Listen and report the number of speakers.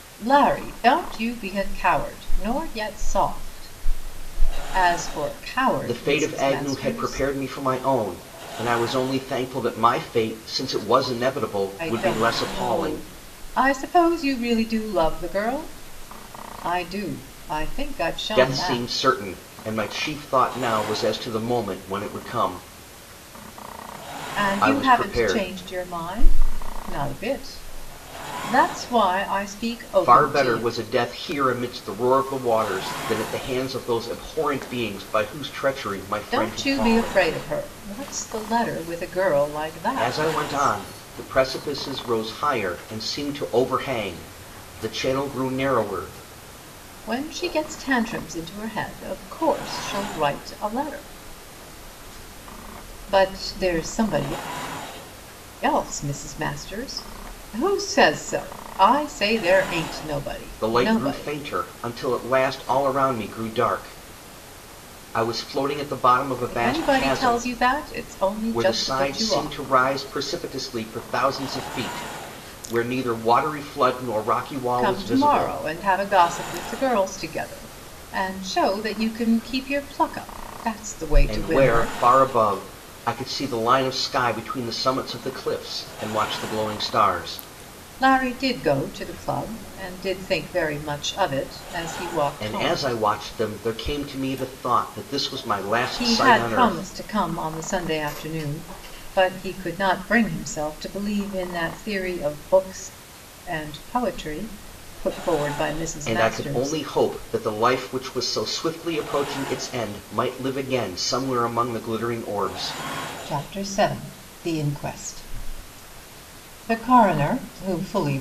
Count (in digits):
2